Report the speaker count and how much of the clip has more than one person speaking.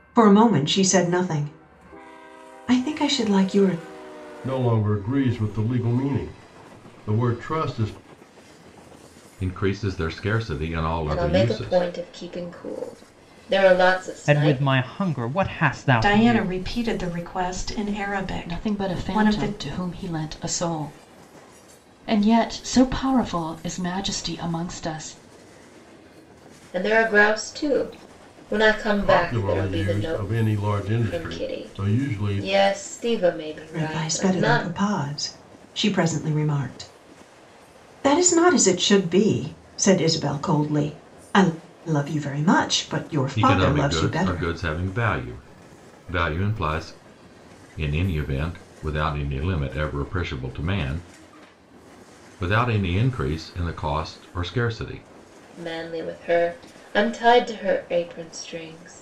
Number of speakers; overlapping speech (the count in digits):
7, about 13%